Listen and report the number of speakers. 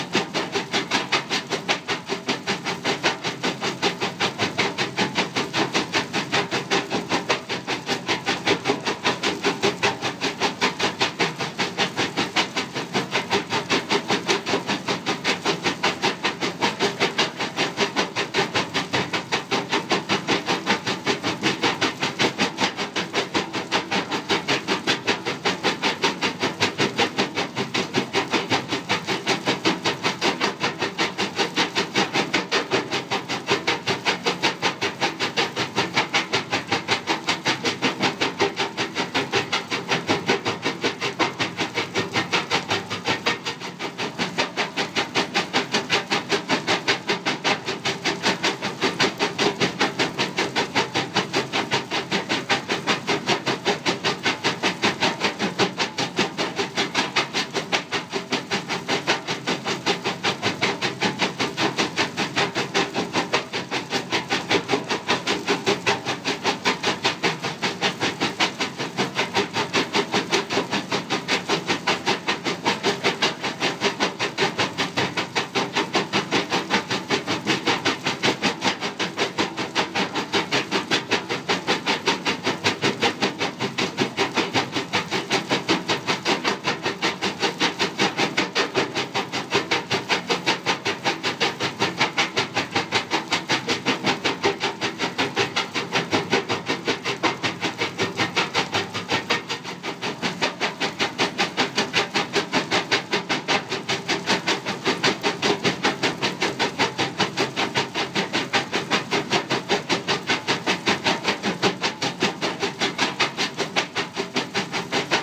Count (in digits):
0